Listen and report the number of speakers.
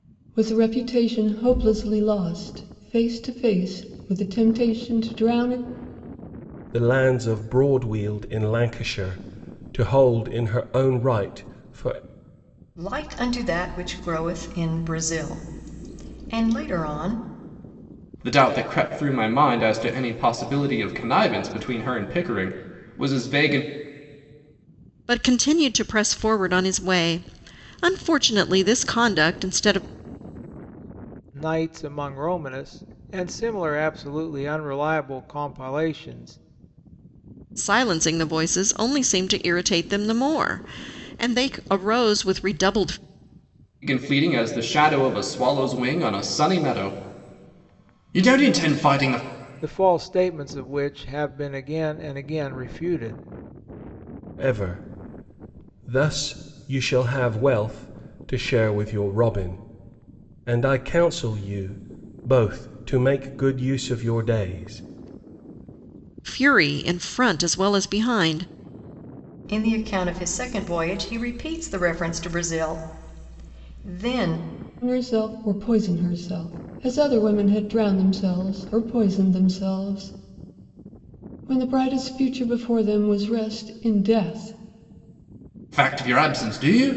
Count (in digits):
6